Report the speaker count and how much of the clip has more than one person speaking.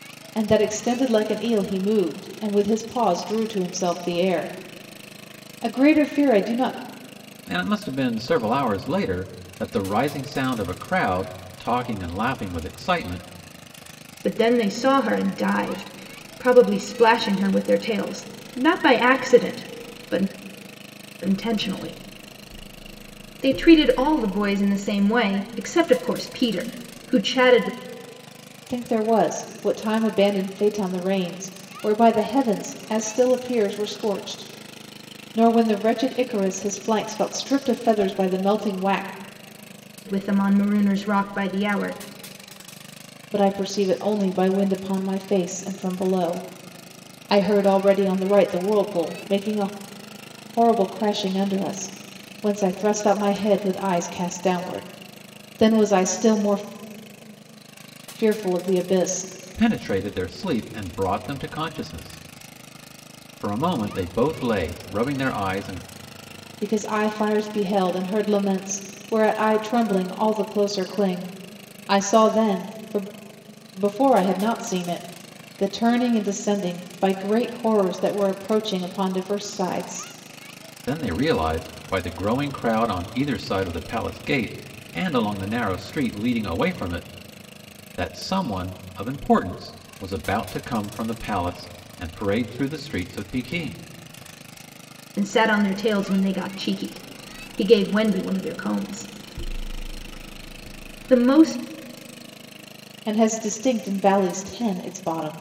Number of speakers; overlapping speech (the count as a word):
three, no overlap